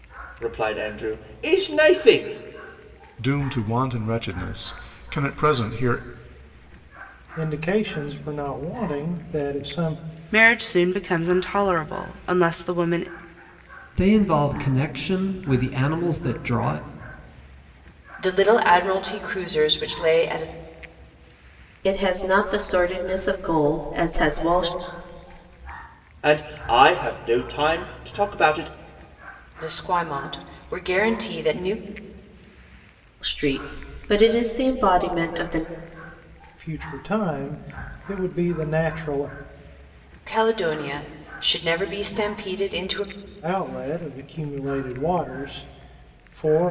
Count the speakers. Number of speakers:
seven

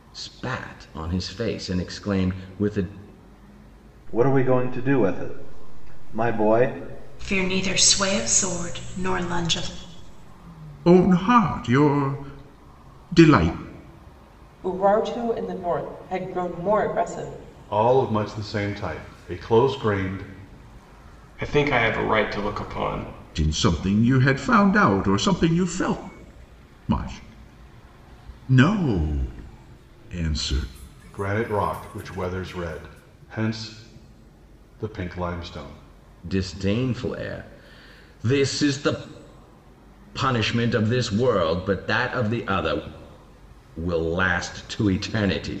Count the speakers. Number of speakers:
seven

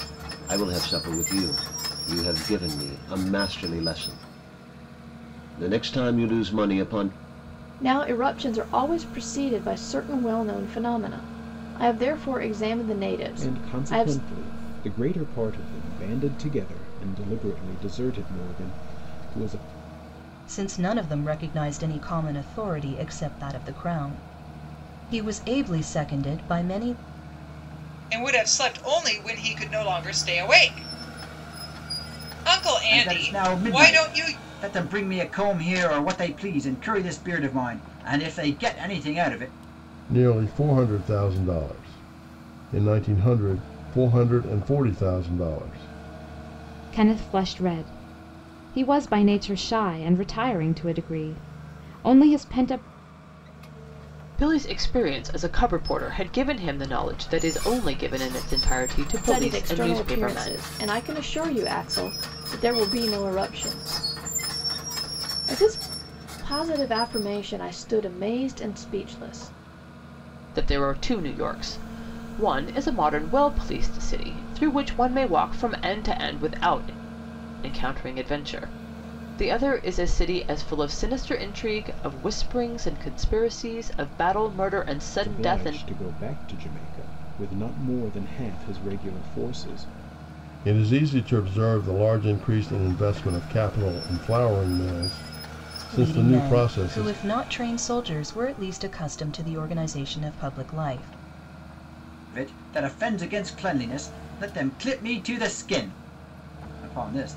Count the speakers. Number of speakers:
nine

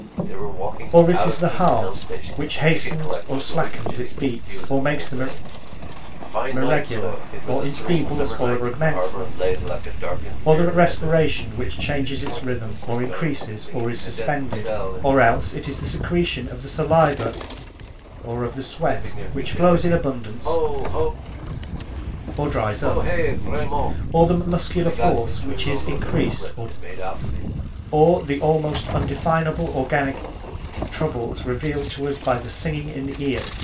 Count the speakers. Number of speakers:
two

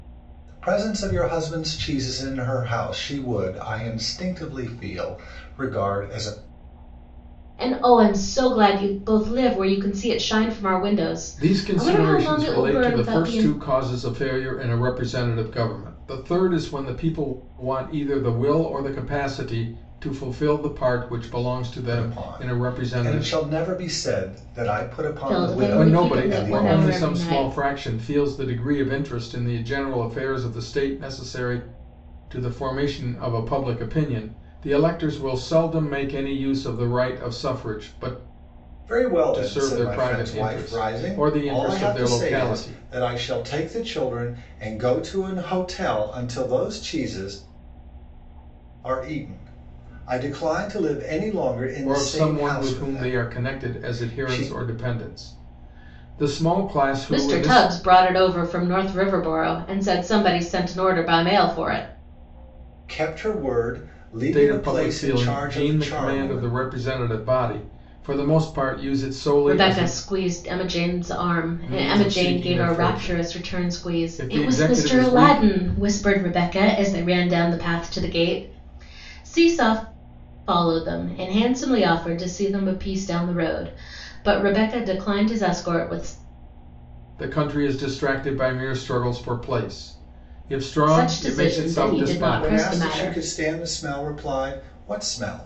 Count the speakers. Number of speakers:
three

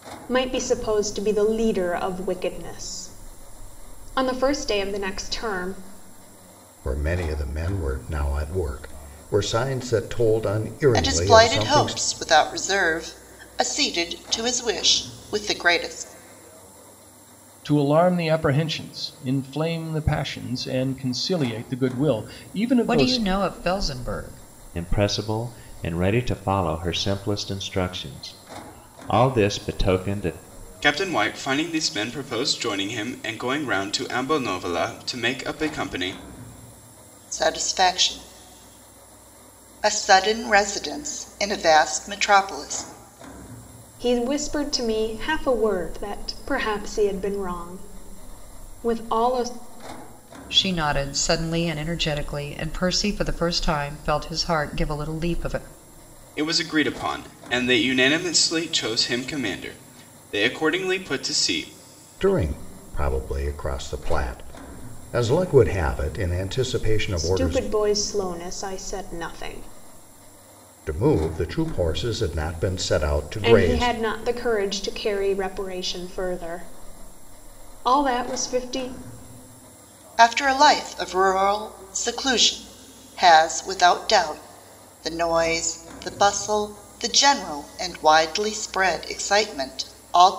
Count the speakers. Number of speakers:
seven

